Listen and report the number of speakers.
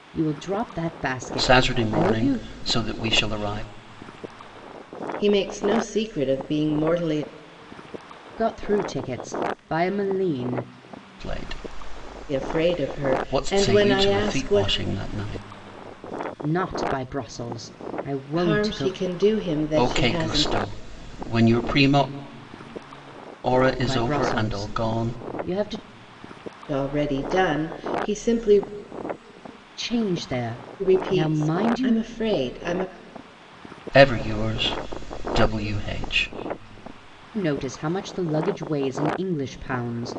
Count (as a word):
three